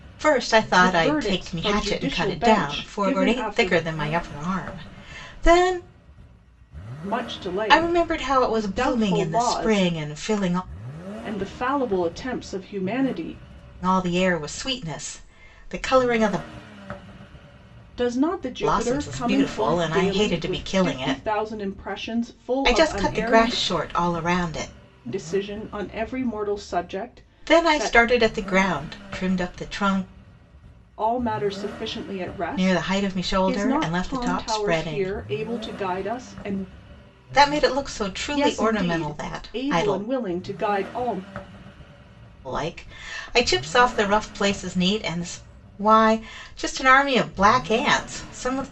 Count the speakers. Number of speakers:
two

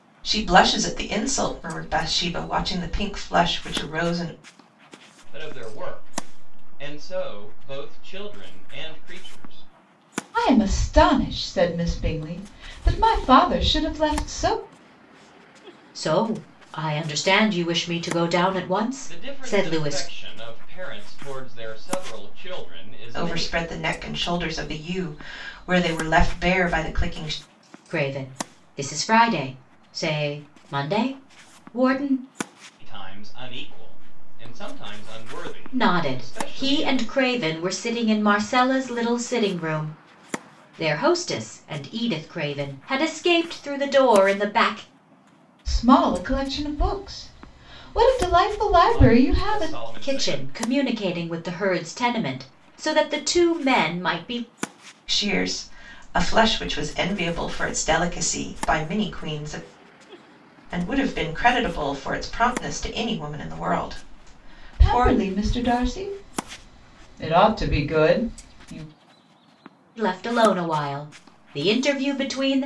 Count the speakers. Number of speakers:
four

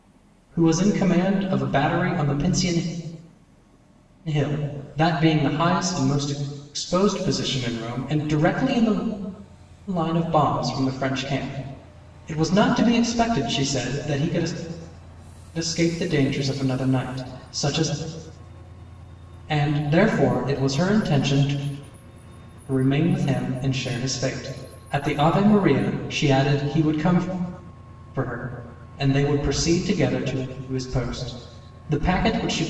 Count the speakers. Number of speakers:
one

